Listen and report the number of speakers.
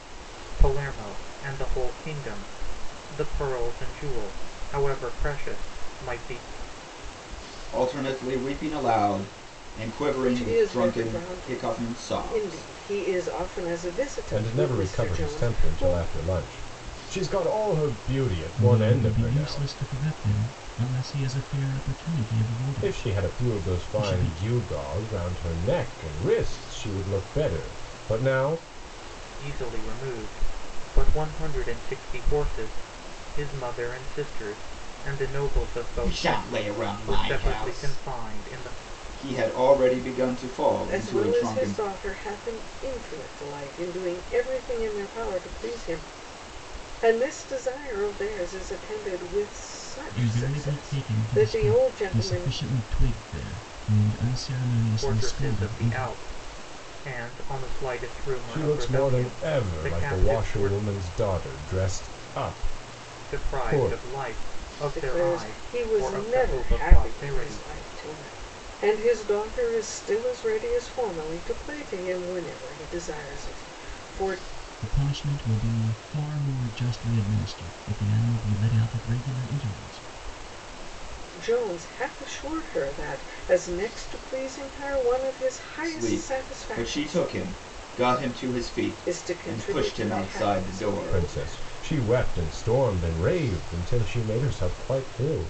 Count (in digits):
5